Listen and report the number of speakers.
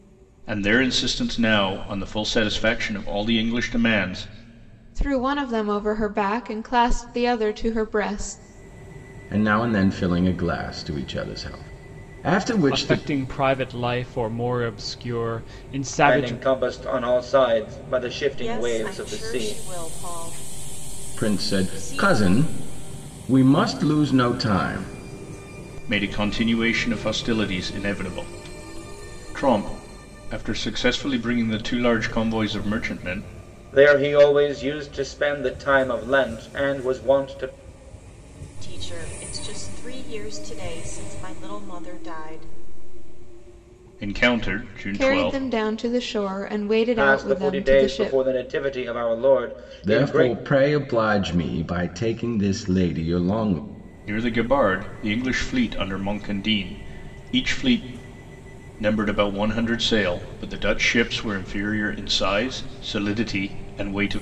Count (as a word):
six